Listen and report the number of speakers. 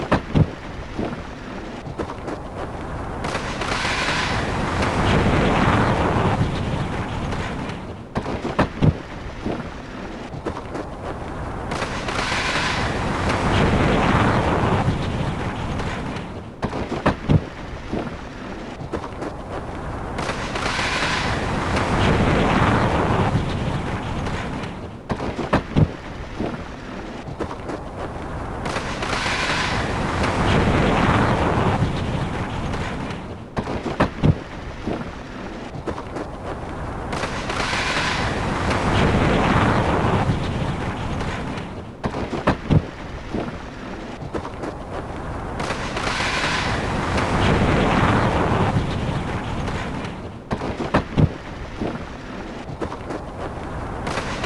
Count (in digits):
0